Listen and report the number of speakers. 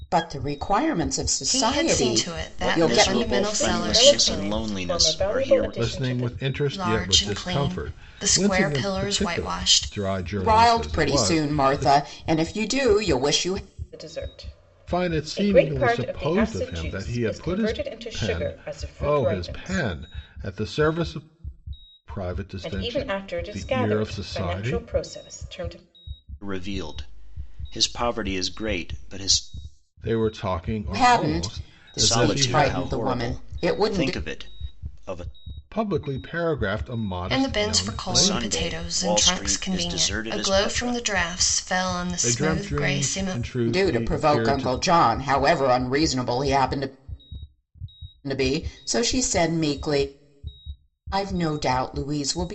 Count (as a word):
five